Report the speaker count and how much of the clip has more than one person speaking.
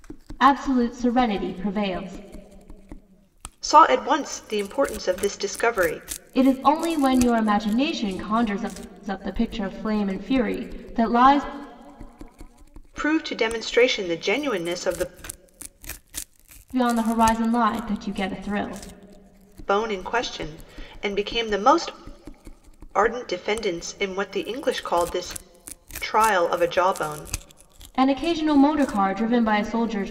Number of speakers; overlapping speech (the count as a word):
two, no overlap